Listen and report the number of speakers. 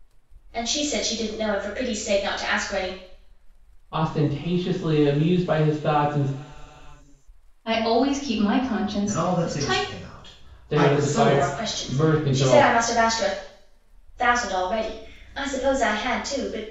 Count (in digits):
4